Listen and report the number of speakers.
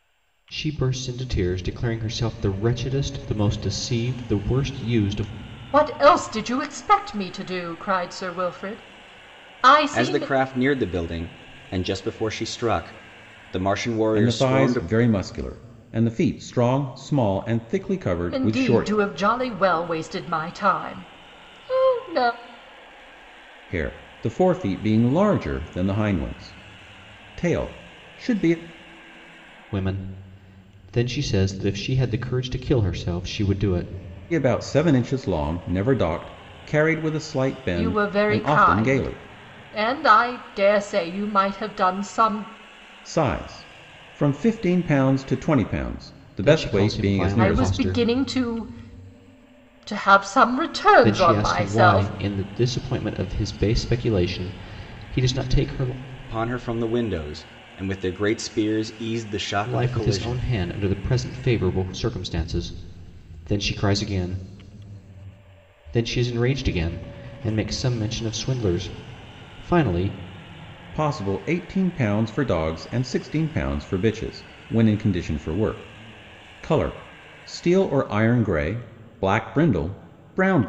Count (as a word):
four